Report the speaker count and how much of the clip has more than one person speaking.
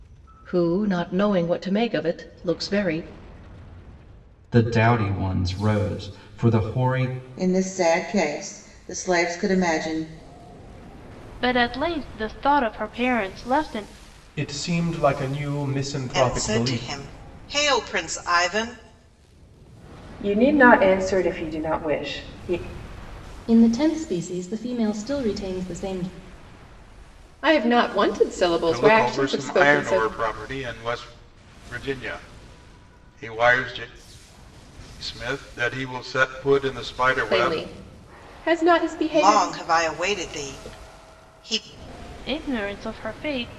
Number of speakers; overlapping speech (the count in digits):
10, about 7%